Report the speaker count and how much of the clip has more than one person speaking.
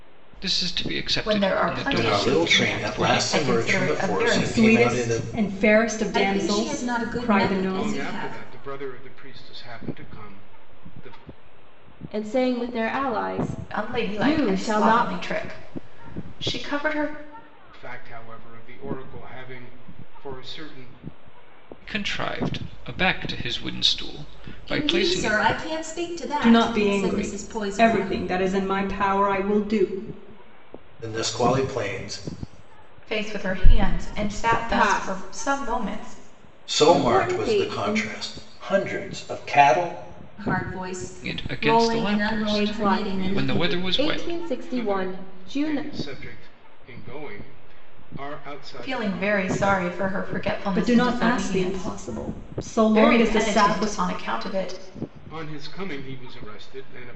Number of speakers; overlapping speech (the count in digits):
7, about 38%